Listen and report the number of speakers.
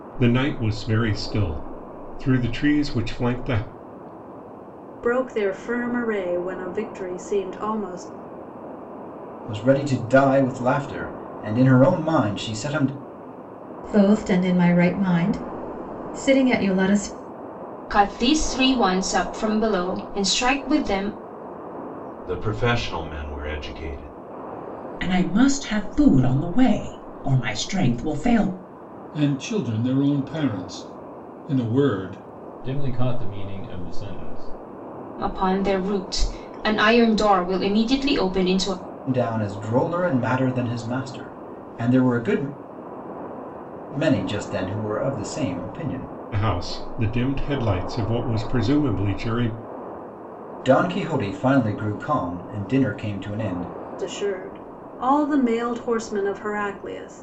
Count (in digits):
9